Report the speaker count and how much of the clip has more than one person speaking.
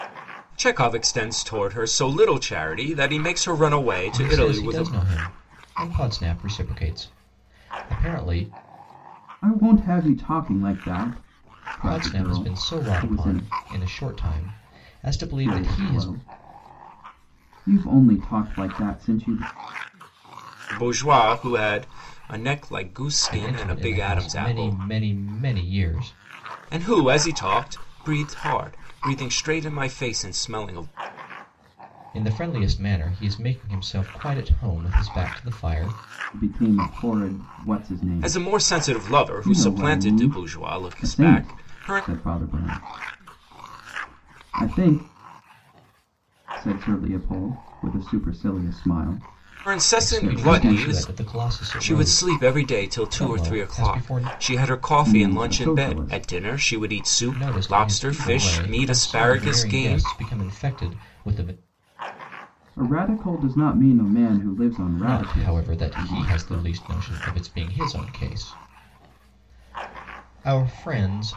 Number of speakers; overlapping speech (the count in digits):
3, about 25%